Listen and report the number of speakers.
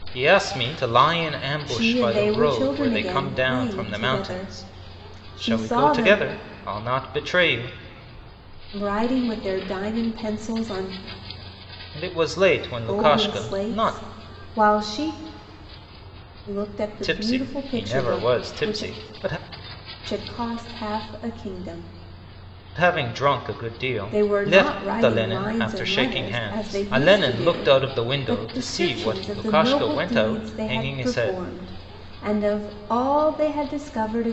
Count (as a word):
two